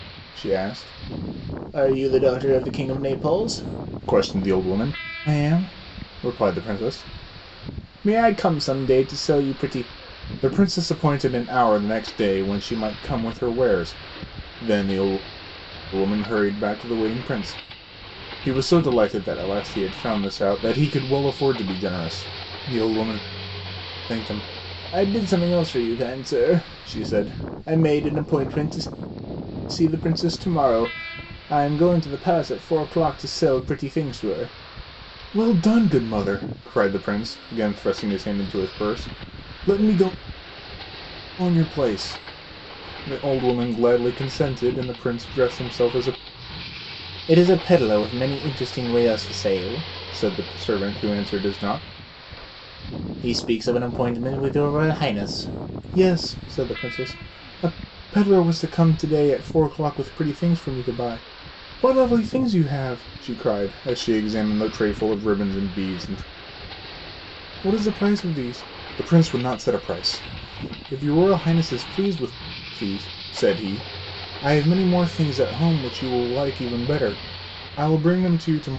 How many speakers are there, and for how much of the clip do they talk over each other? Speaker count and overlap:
1, no overlap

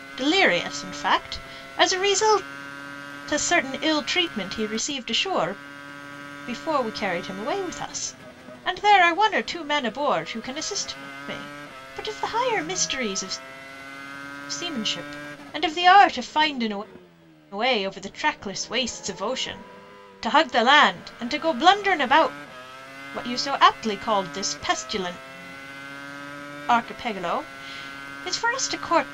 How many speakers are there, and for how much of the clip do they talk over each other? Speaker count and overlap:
1, no overlap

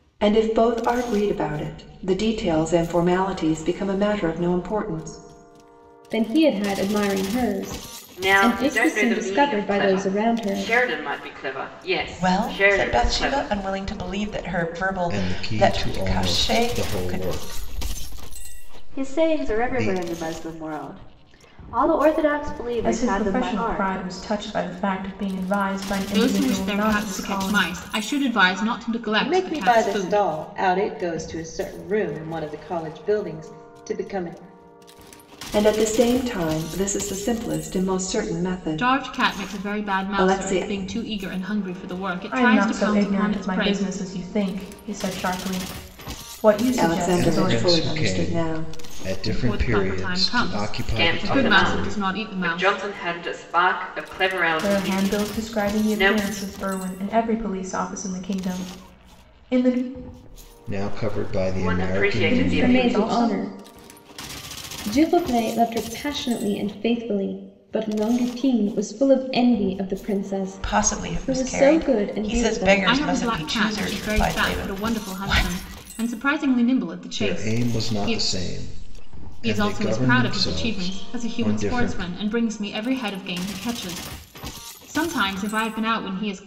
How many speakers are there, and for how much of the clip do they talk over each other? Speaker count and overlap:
9, about 39%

